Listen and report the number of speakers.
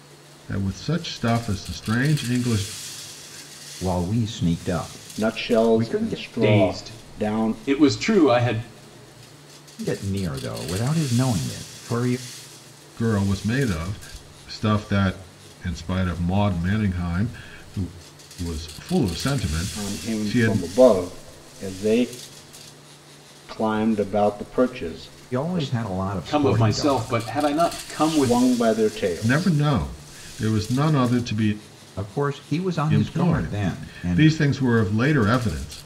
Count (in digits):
4